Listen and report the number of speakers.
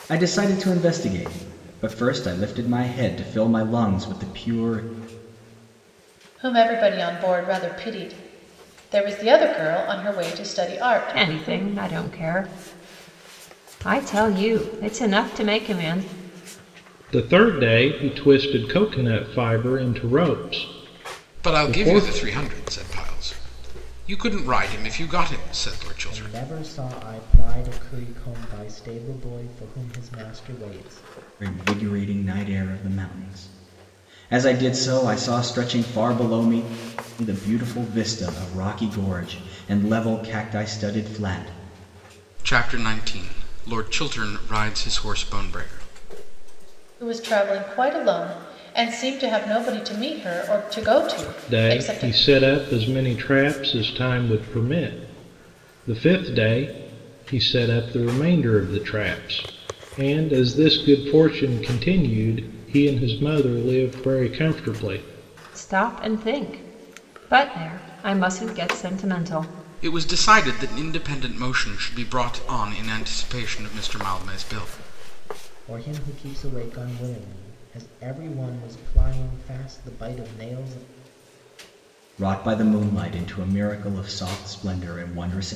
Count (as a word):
six